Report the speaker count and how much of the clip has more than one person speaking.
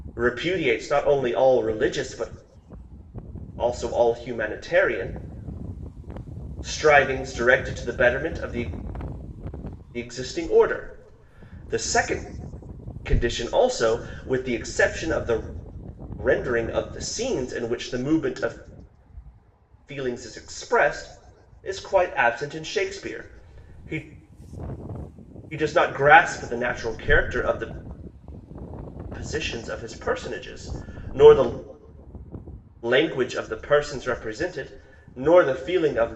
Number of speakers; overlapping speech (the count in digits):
1, no overlap